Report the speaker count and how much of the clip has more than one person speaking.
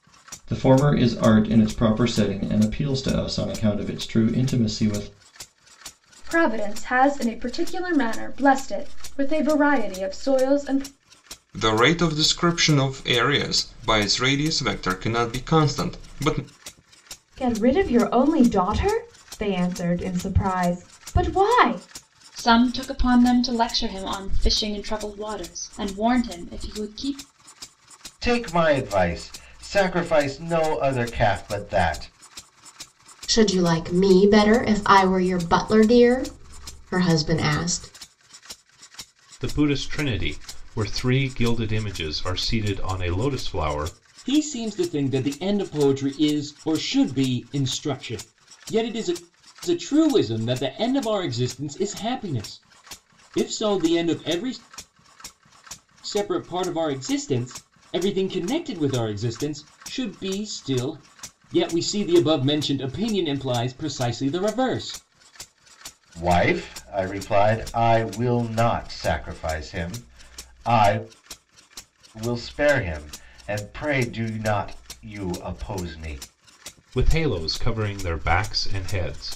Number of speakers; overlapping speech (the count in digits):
9, no overlap